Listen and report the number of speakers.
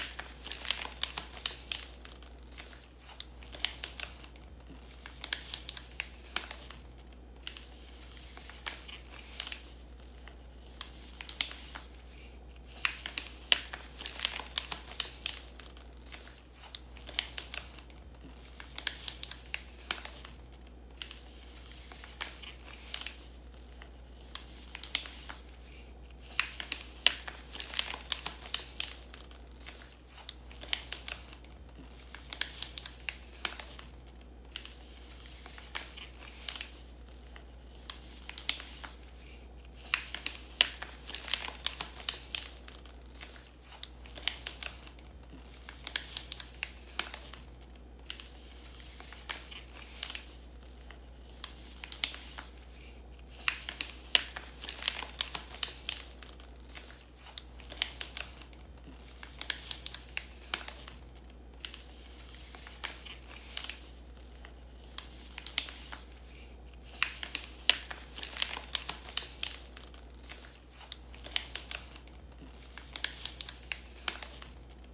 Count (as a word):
zero